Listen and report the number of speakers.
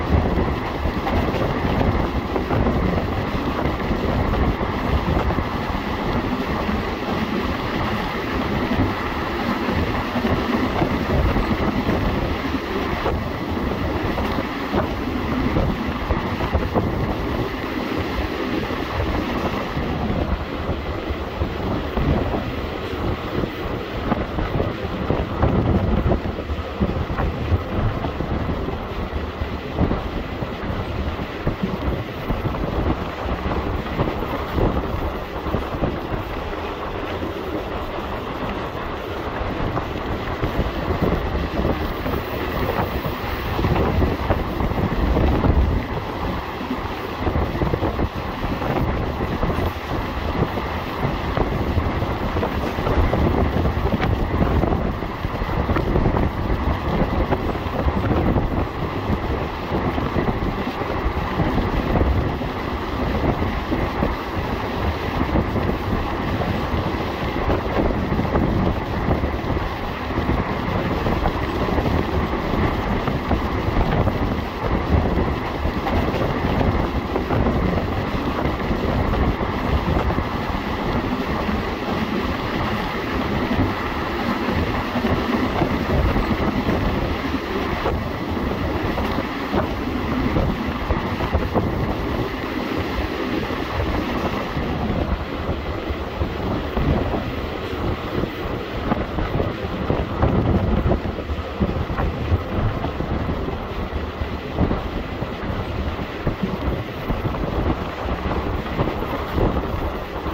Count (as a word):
zero